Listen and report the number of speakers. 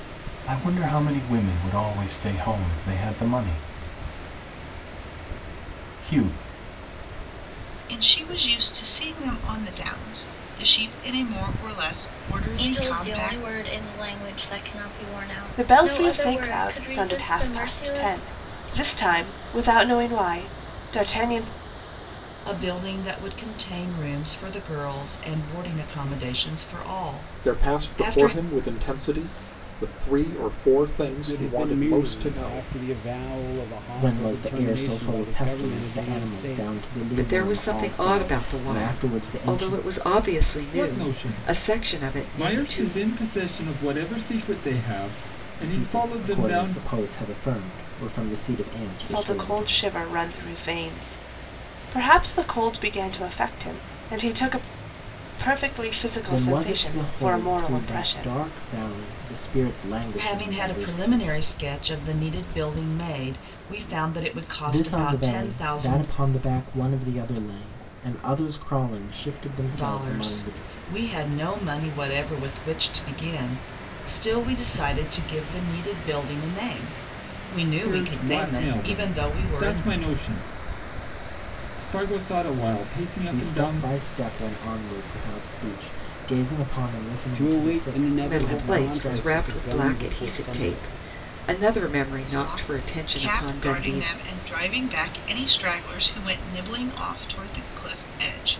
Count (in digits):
10